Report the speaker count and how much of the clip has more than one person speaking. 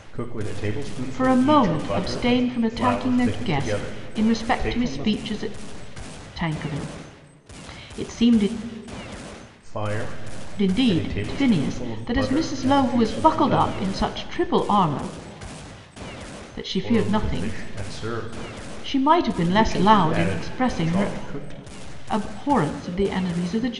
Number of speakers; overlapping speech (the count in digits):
2, about 42%